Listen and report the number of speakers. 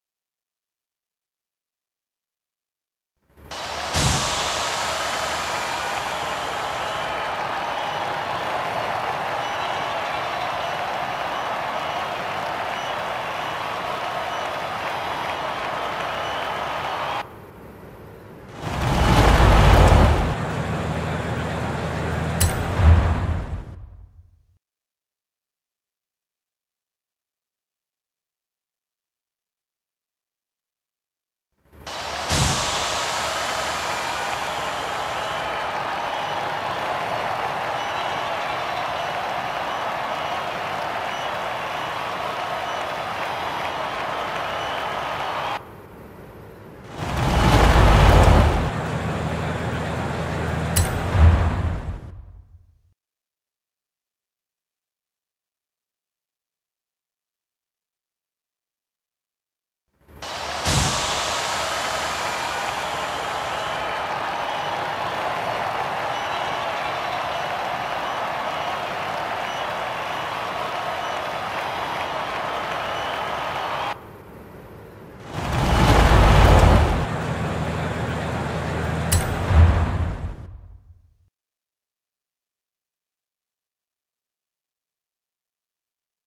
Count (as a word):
zero